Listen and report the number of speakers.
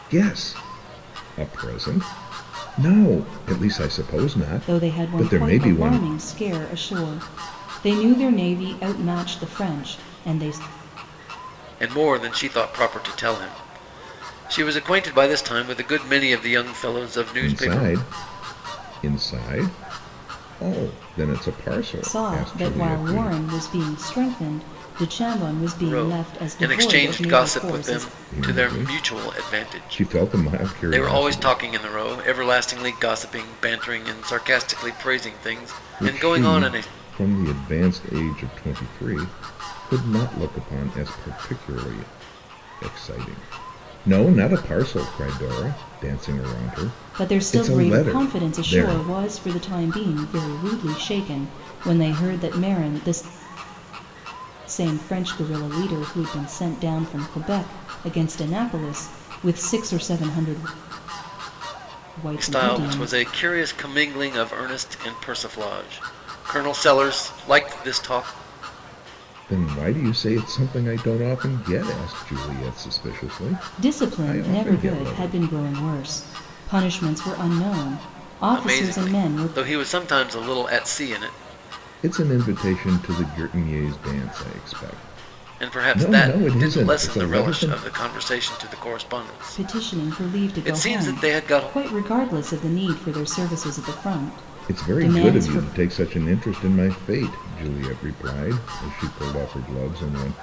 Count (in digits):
3